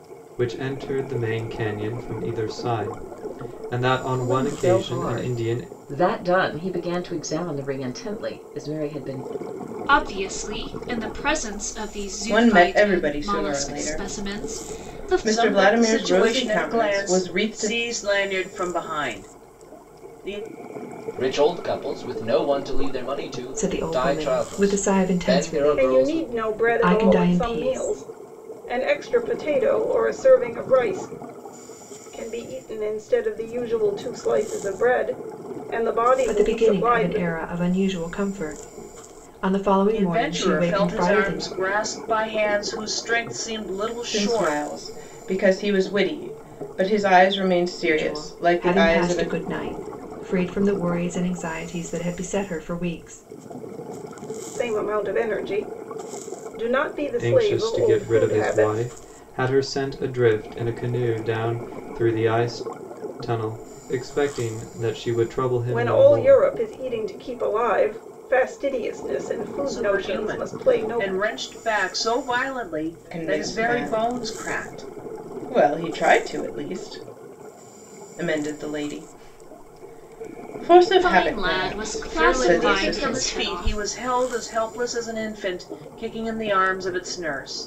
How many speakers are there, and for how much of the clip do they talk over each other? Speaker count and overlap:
8, about 29%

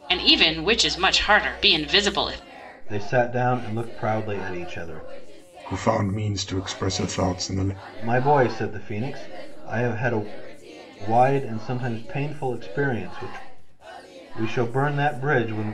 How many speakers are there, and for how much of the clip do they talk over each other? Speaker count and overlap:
3, no overlap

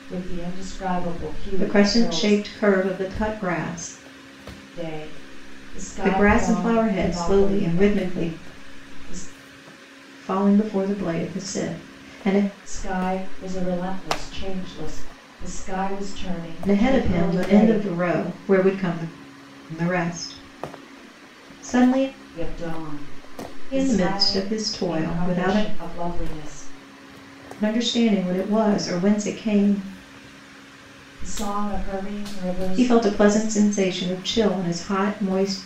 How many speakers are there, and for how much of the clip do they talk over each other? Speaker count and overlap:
2, about 19%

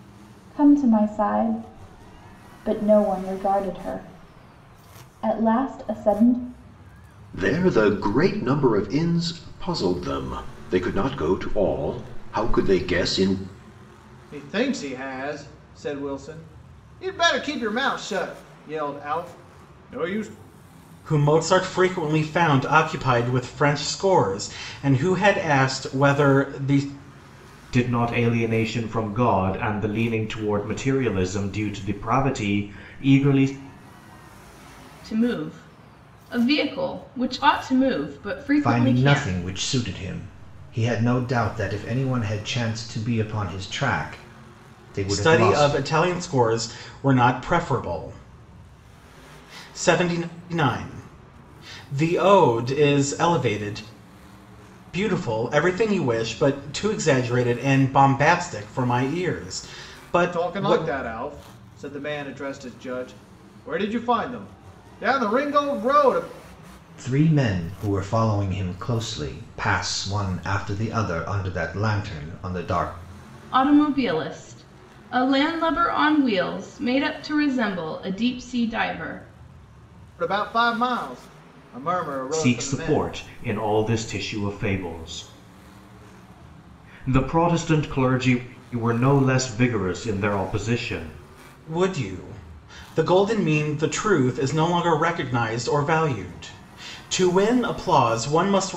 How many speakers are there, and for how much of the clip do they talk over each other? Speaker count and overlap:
7, about 3%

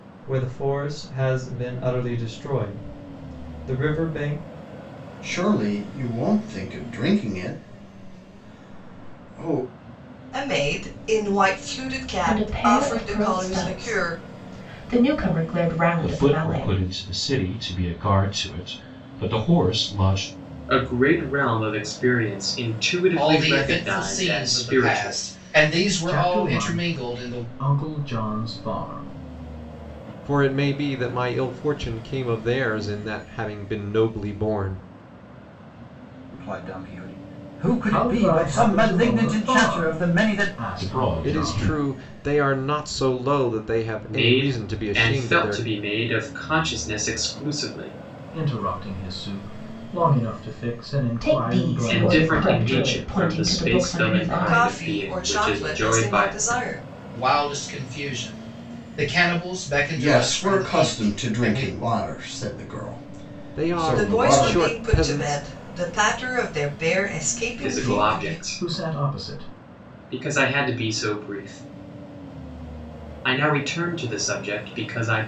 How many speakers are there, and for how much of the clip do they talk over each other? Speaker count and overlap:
10, about 29%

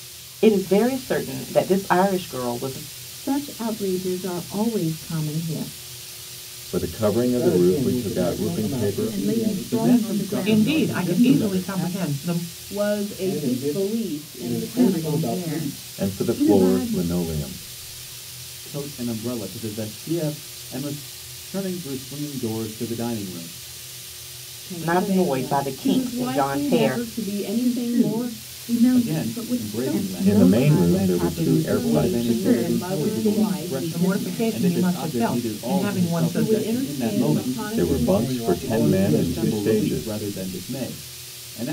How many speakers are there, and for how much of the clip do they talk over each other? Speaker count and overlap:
8, about 54%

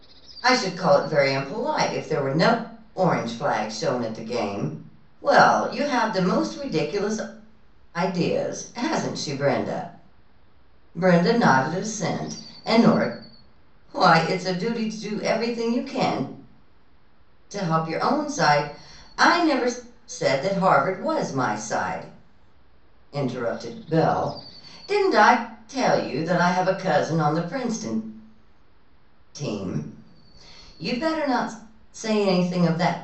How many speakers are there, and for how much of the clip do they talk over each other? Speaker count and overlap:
1, no overlap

